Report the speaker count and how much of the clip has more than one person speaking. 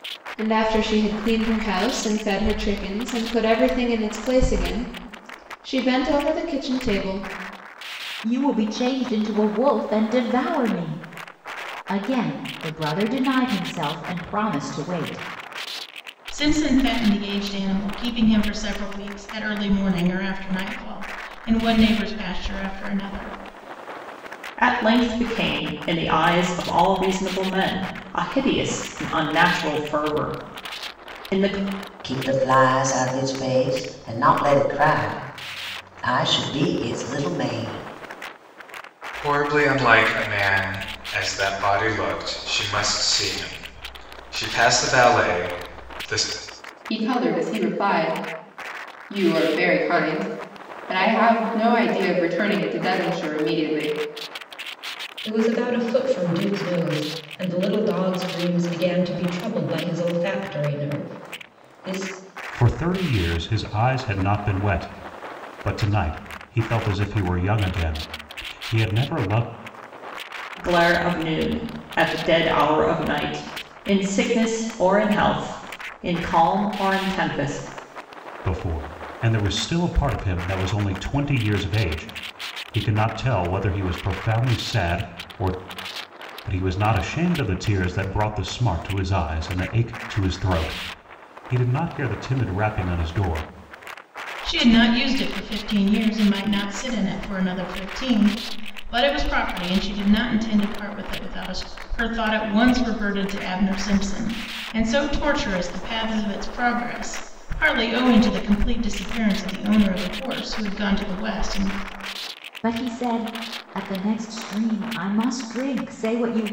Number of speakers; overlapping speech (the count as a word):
nine, no overlap